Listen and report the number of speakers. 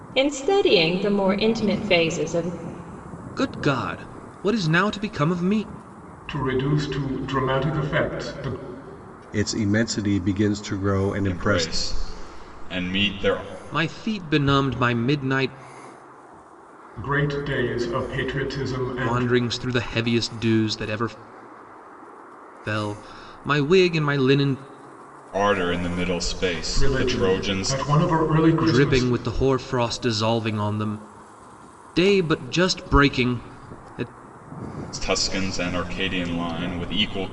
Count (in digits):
5